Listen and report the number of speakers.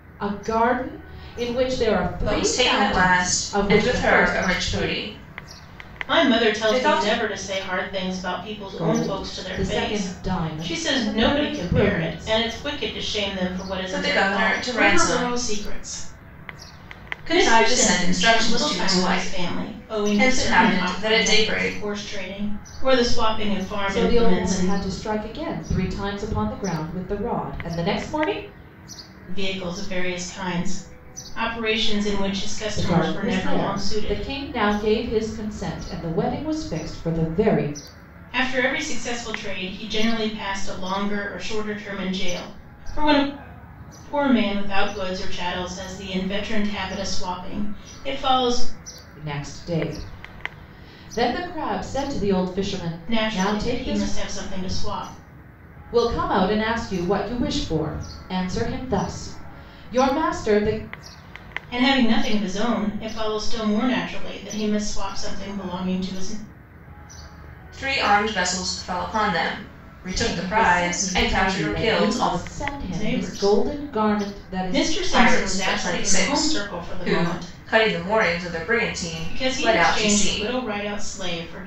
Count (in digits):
3